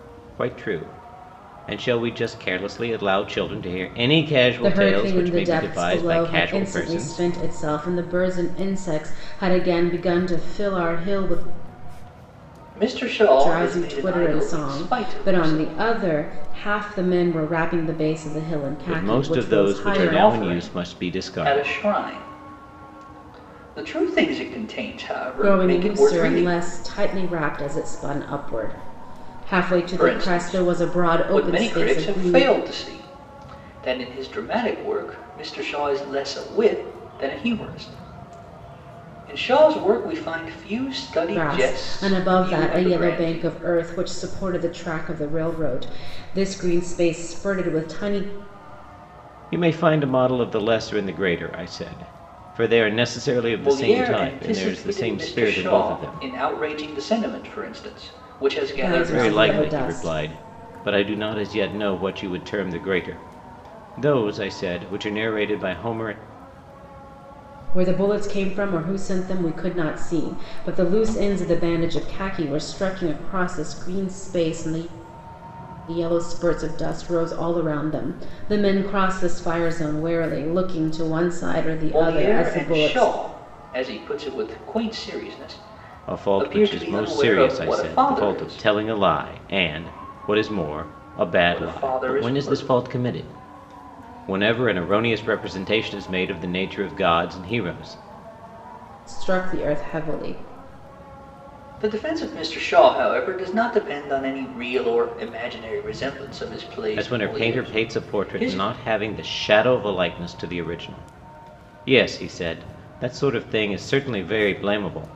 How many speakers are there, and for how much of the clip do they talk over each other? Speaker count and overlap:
three, about 22%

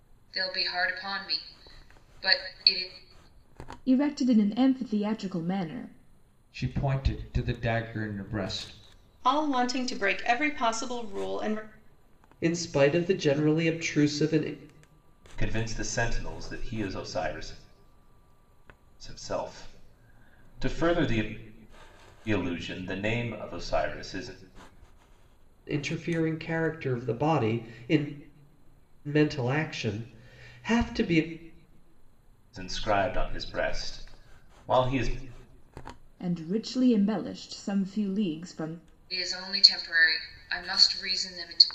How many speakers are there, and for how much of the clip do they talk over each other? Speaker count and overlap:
six, no overlap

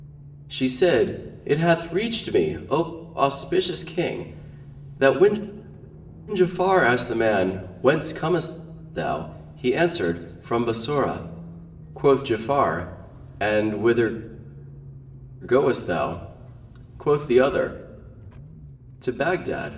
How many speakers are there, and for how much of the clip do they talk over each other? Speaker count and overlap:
one, no overlap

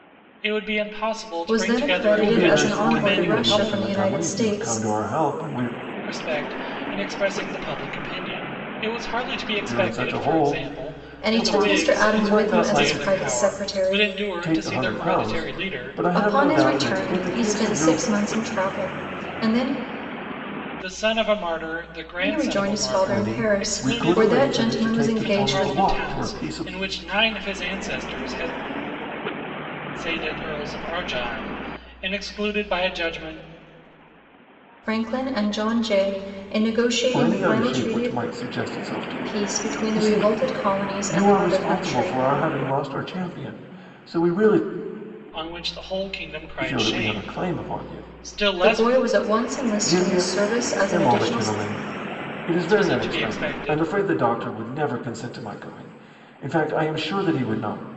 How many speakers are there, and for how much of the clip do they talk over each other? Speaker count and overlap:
three, about 42%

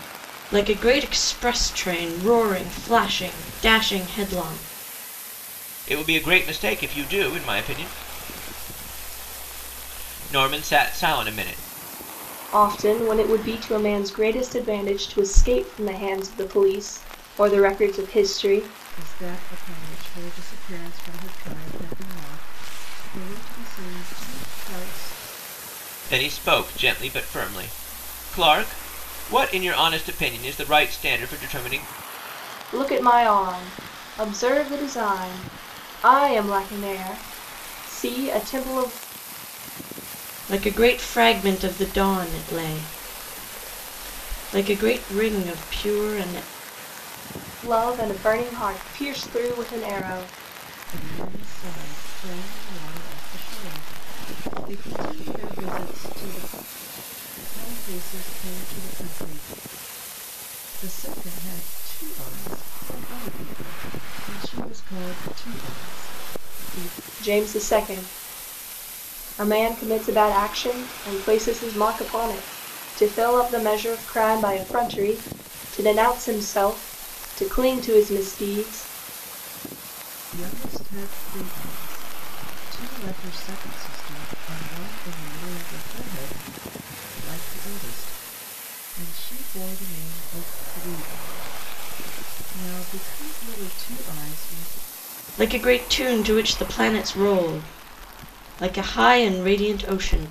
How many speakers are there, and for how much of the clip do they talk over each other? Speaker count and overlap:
four, no overlap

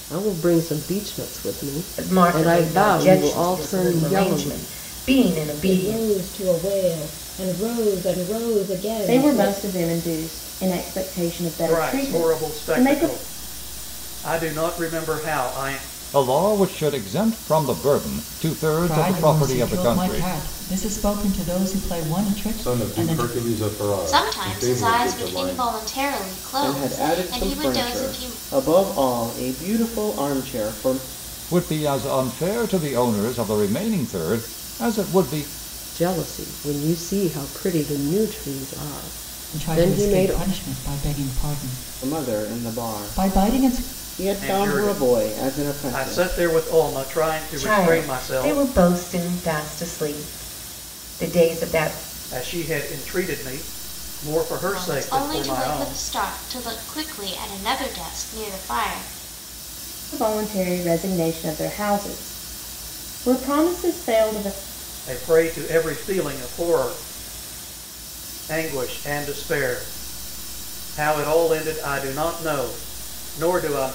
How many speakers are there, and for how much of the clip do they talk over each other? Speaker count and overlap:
ten, about 25%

